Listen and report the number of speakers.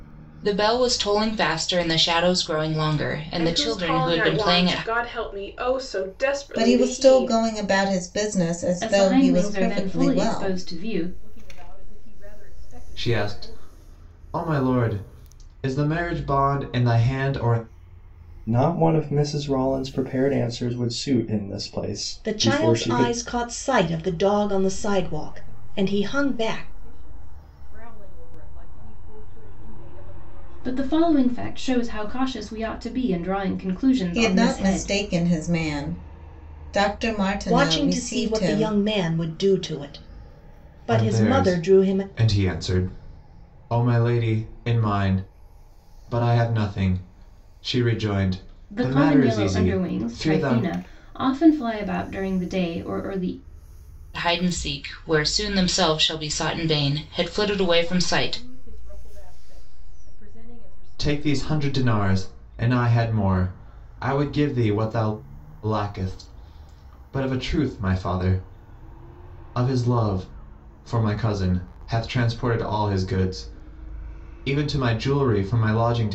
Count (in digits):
8